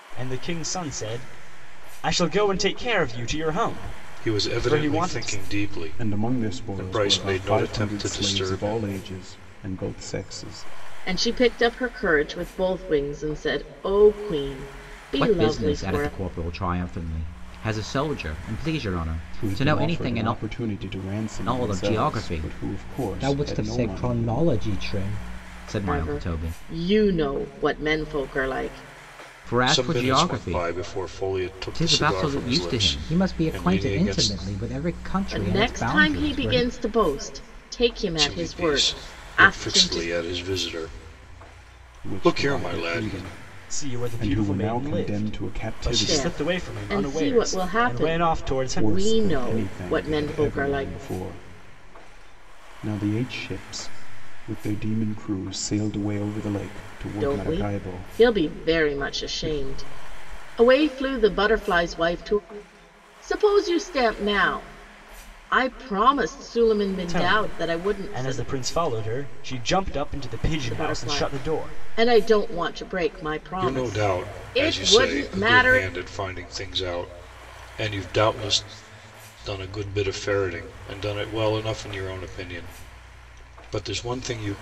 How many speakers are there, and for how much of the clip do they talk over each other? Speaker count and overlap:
5, about 39%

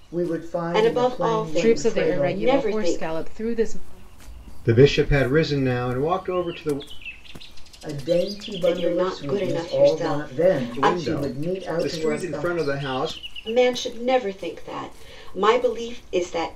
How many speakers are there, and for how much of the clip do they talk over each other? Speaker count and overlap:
4, about 39%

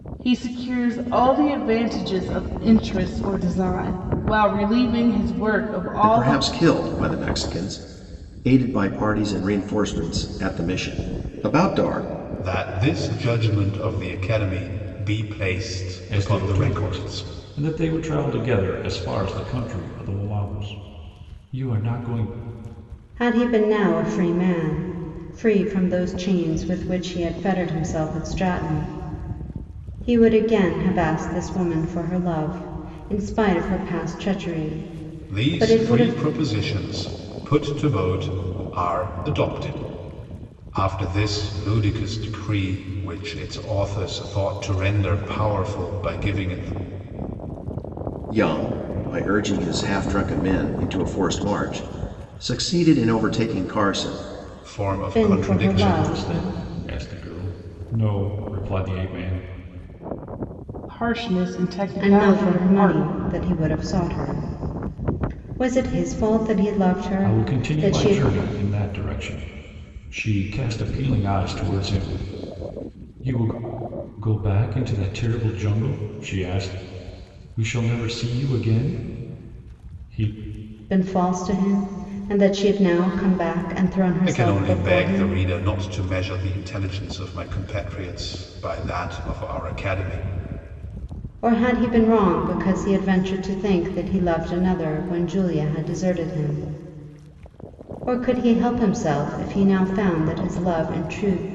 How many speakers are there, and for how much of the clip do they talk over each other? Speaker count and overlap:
5, about 7%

